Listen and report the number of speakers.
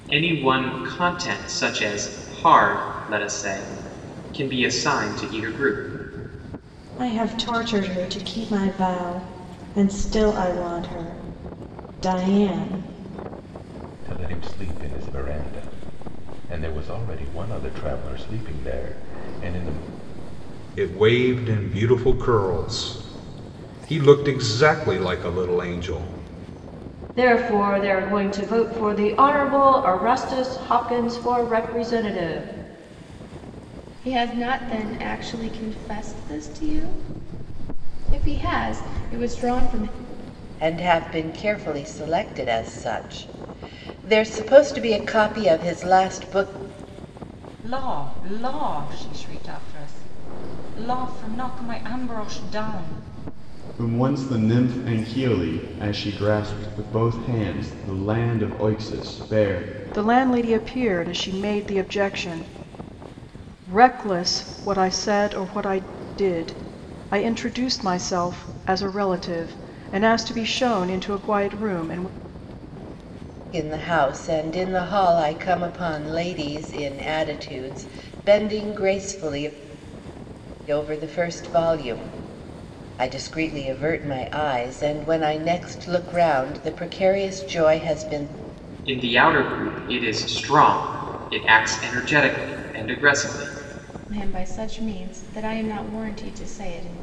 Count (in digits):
10